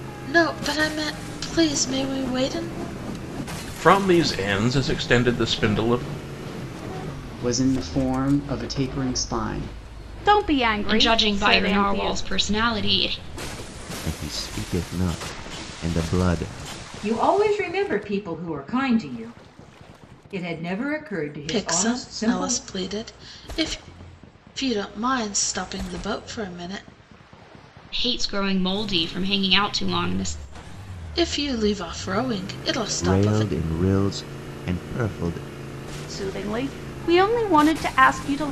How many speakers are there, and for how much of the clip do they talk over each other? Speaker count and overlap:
7, about 8%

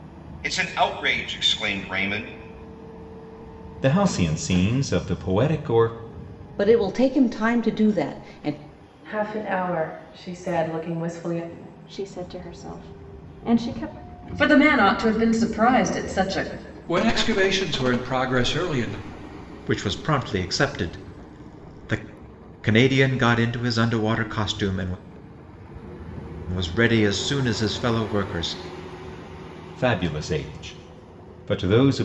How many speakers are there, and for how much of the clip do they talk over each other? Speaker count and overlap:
8, no overlap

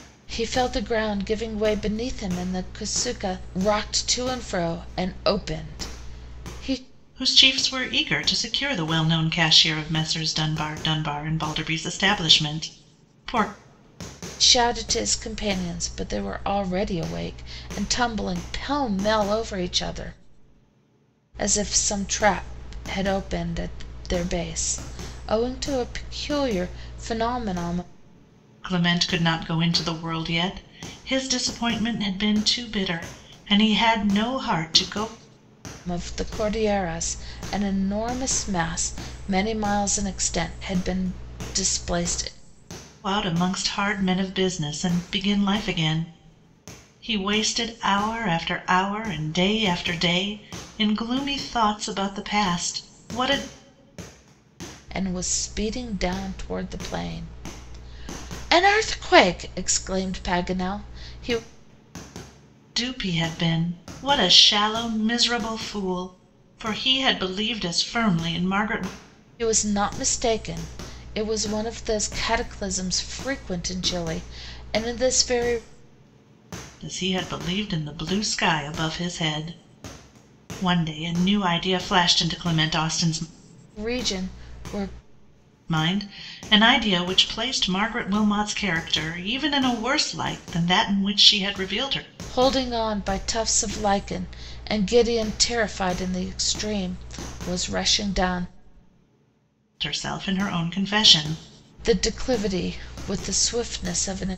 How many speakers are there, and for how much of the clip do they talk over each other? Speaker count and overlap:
2, no overlap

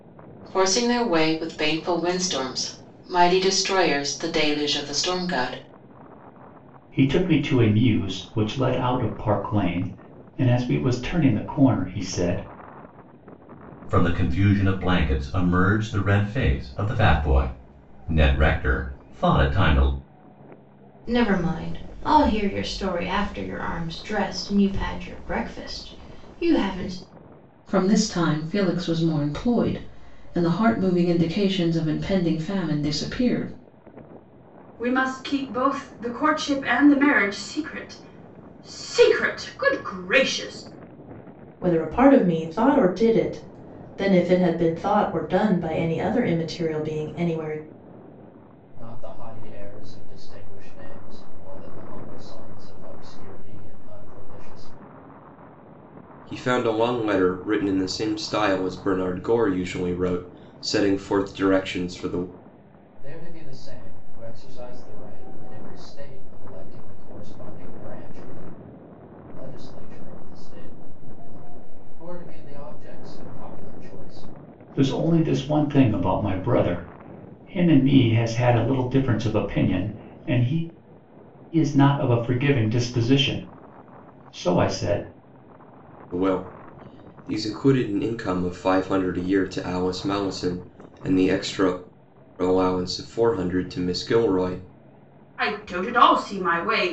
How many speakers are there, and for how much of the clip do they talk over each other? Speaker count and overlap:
9, no overlap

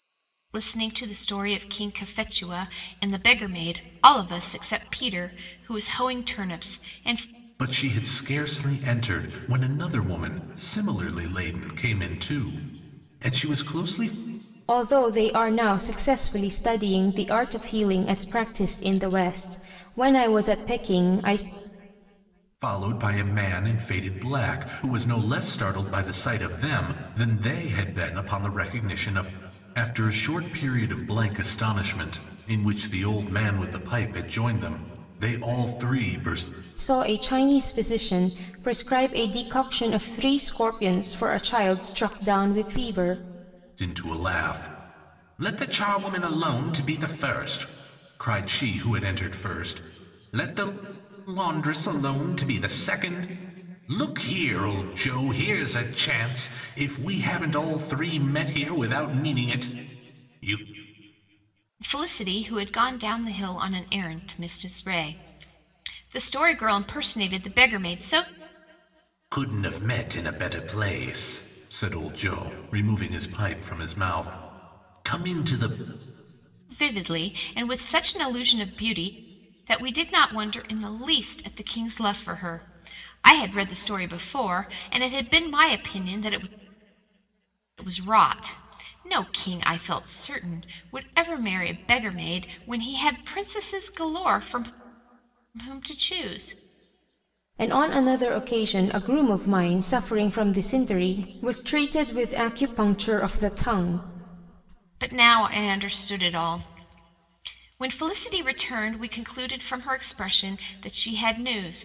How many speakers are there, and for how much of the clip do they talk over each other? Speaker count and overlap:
3, no overlap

